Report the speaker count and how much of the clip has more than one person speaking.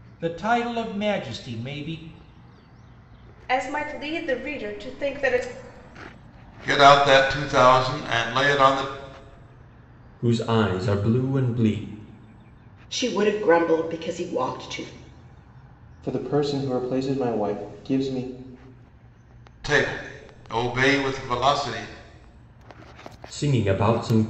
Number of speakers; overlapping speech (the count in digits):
6, no overlap